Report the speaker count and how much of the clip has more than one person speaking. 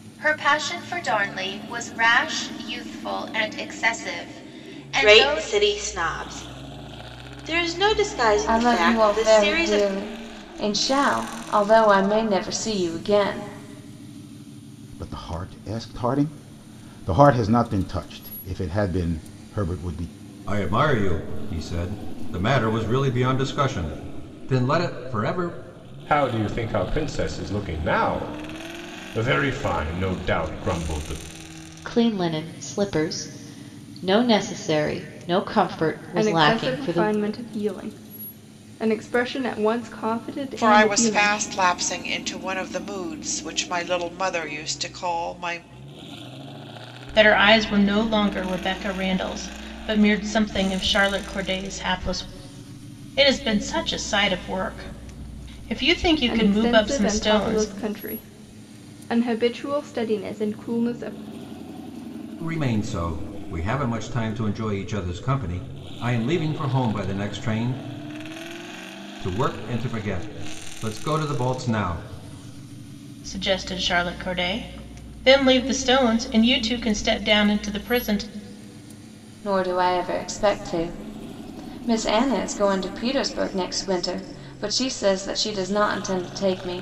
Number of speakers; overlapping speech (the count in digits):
10, about 6%